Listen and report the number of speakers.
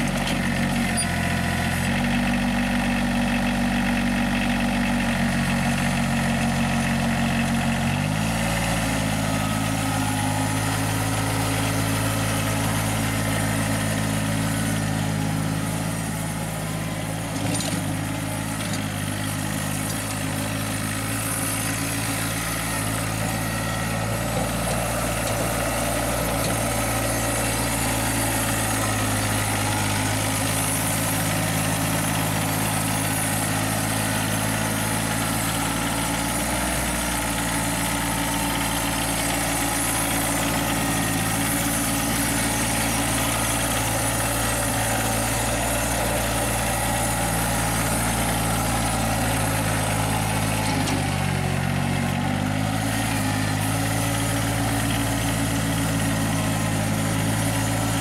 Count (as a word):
zero